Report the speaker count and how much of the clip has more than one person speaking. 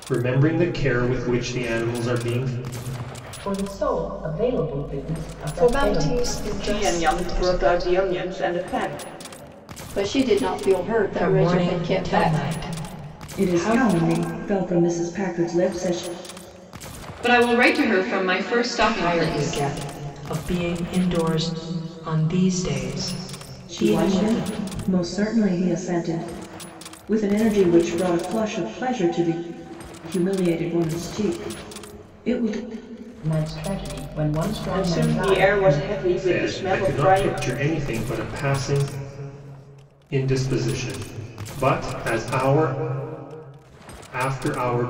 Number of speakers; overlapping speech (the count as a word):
eight, about 18%